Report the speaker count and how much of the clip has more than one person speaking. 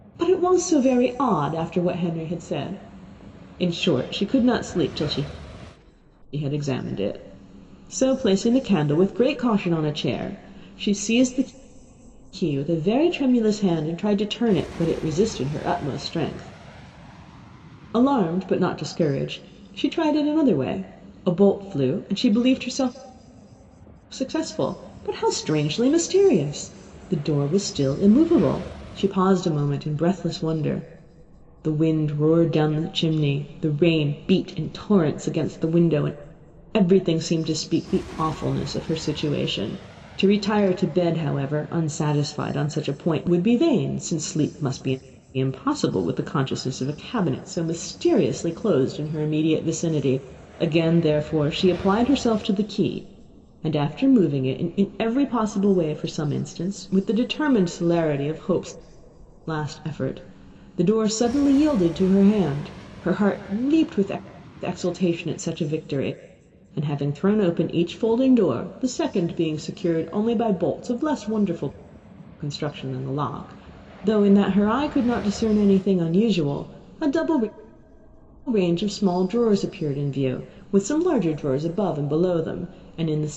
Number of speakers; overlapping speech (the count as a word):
one, no overlap